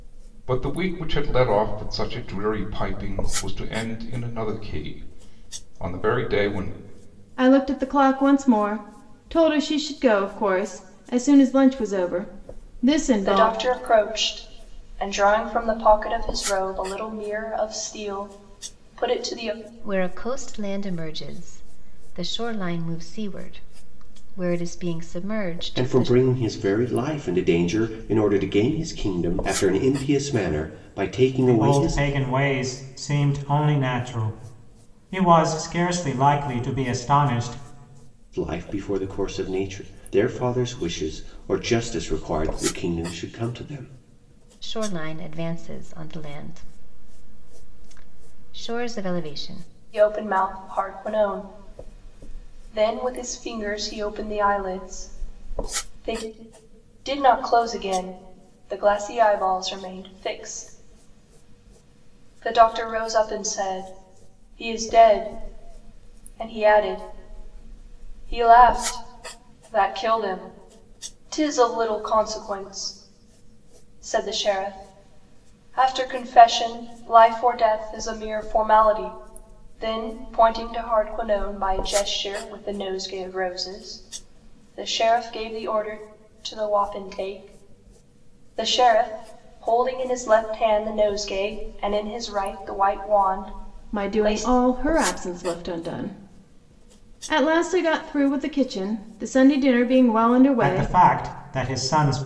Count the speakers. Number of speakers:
6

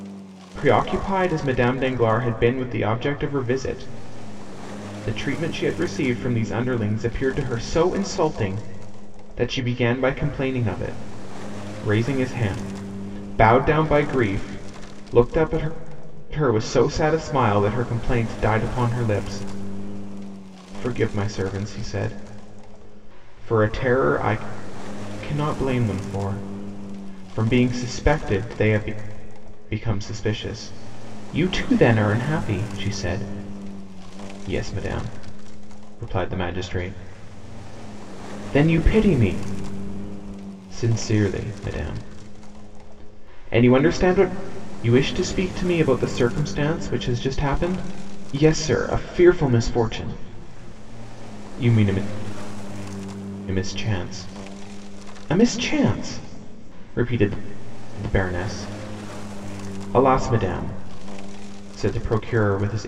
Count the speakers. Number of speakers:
1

